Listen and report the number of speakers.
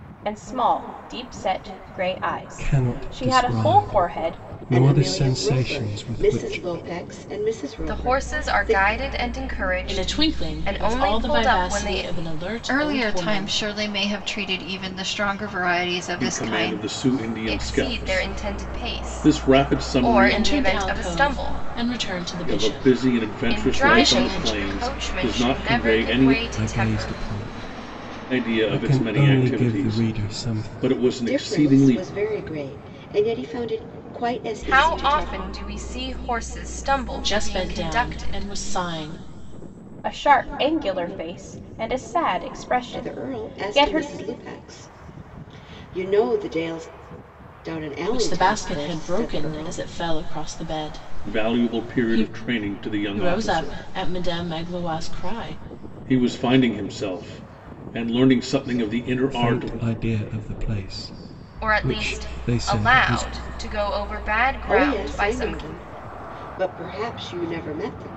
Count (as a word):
seven